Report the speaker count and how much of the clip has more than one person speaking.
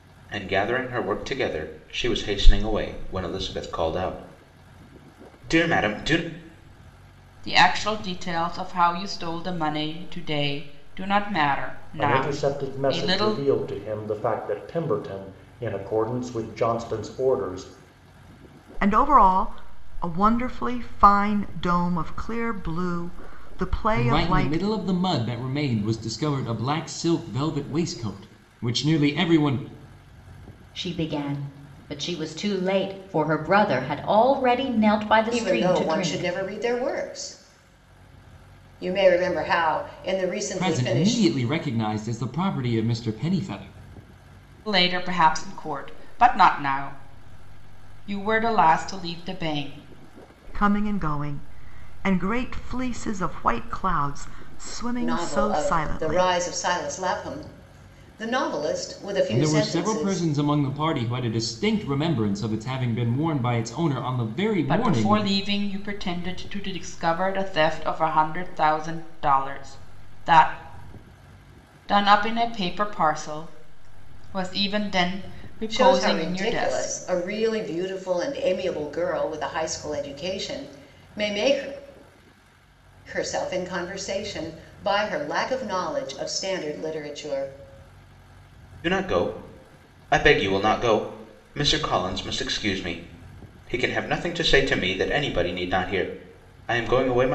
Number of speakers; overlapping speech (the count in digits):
7, about 9%